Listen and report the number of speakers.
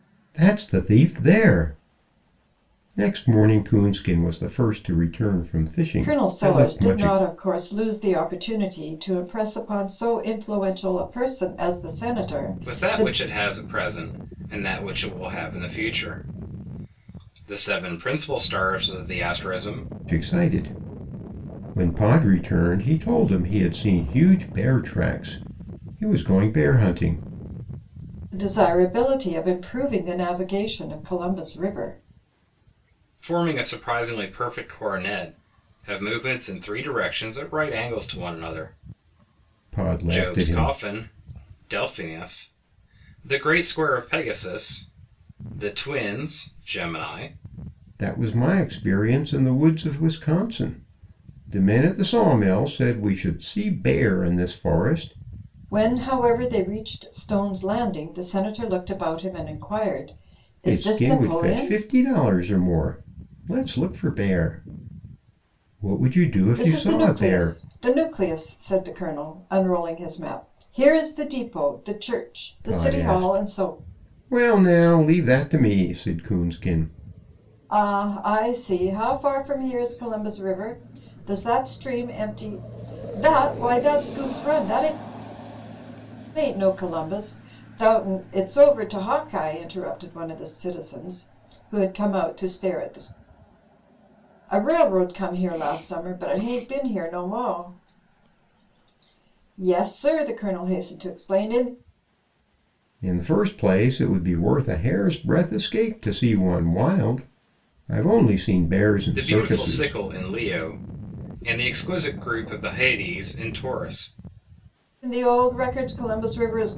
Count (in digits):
3